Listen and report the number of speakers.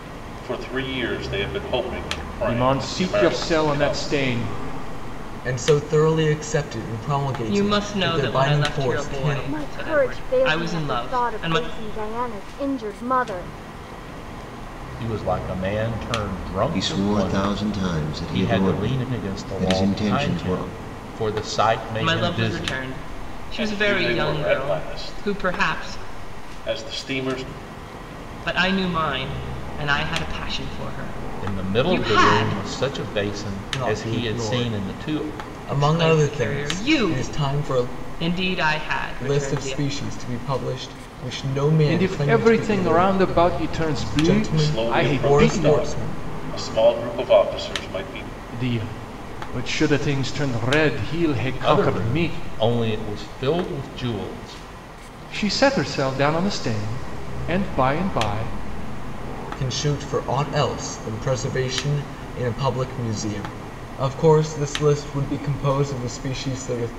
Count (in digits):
7